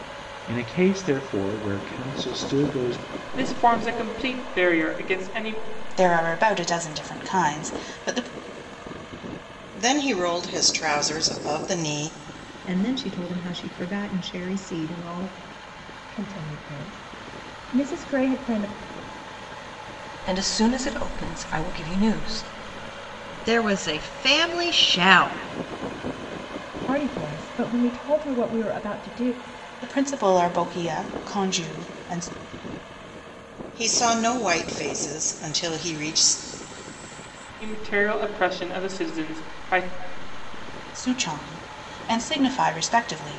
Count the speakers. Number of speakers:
eight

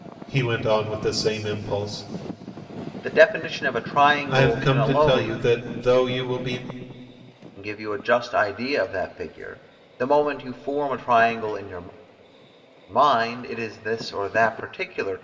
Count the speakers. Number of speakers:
two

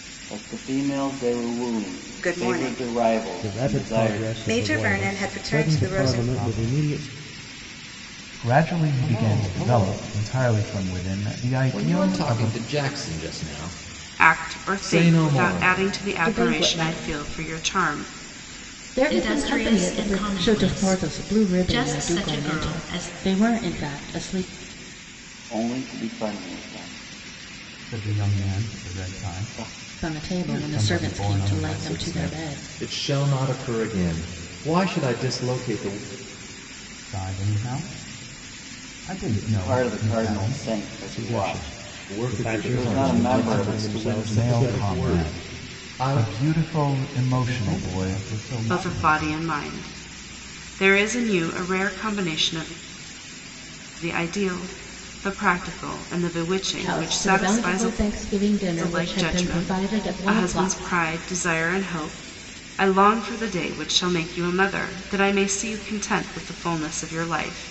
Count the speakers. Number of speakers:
ten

